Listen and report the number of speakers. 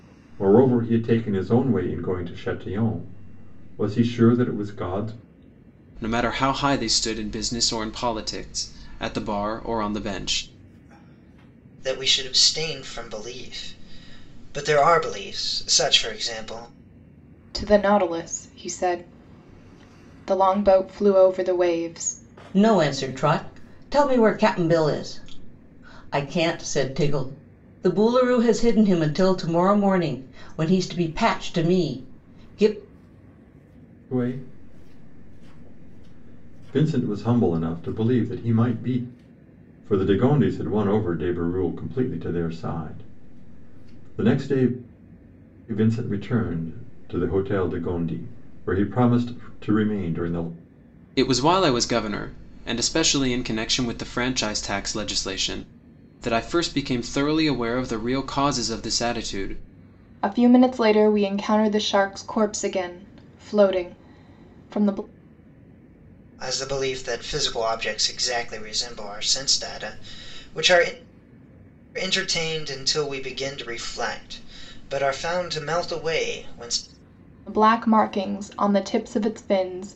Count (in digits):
5